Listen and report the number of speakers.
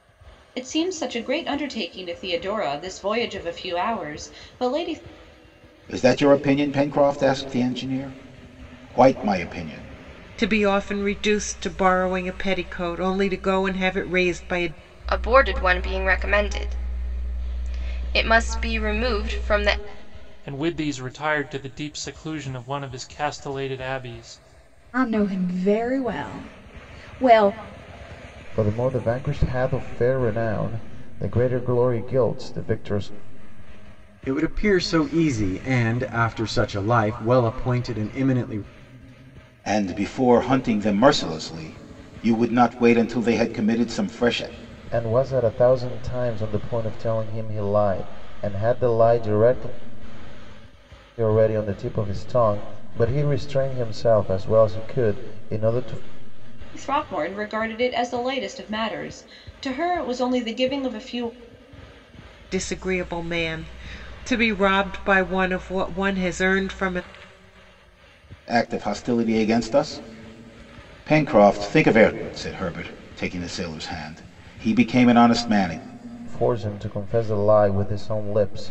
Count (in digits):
8